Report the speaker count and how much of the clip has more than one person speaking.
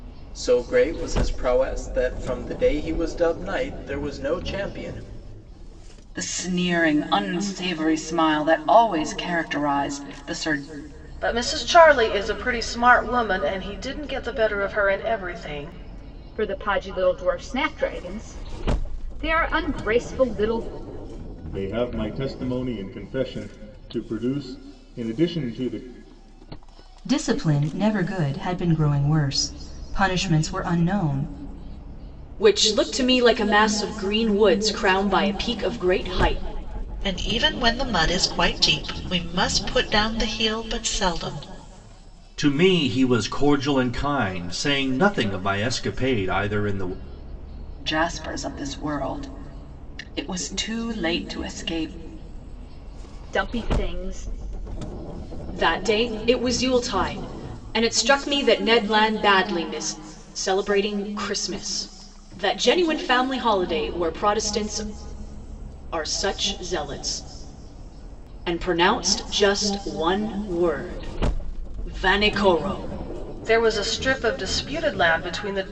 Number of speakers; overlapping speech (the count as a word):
nine, no overlap